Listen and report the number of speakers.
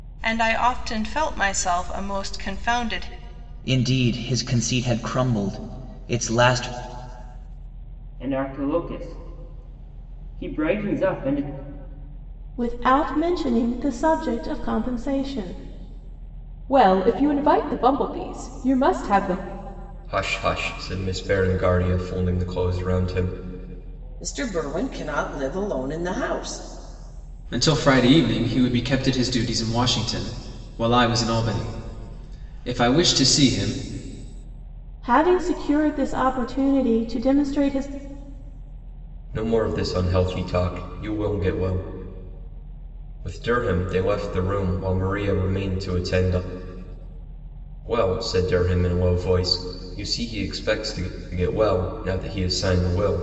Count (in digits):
8